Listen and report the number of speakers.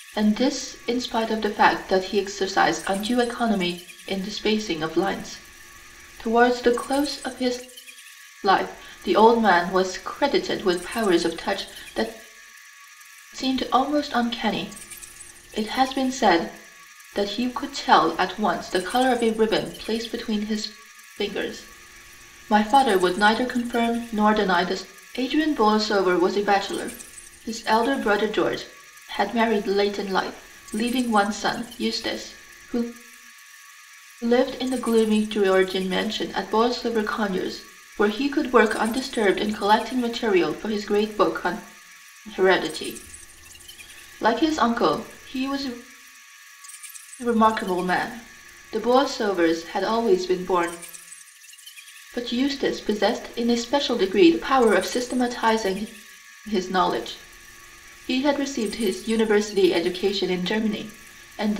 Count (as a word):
one